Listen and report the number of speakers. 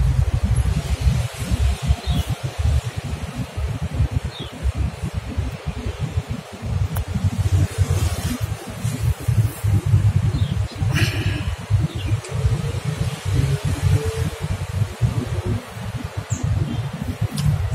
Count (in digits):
0